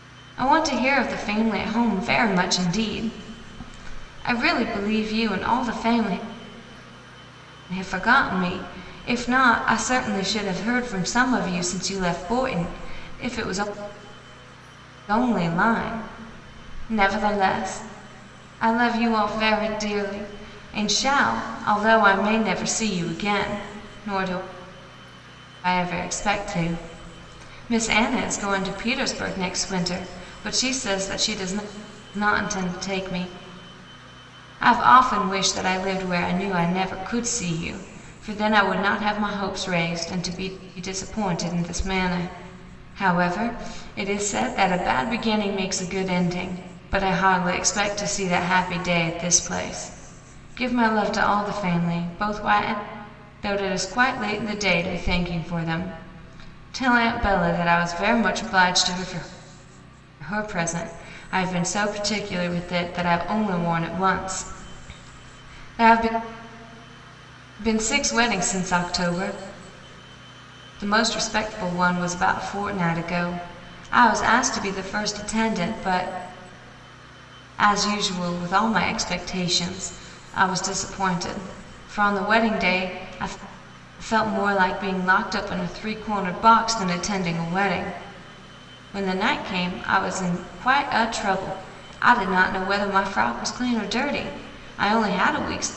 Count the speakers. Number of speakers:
1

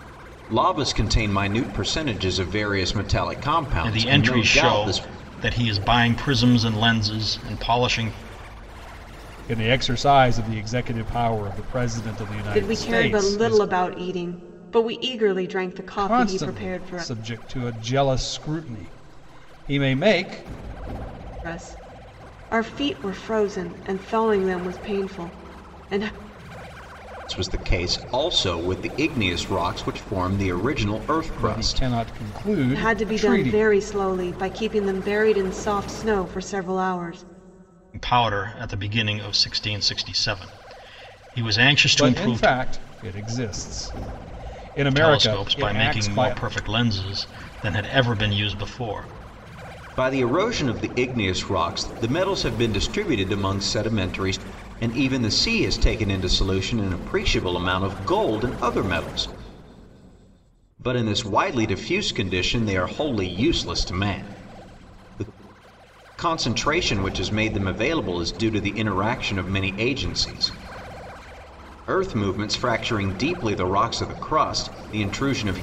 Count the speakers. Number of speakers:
4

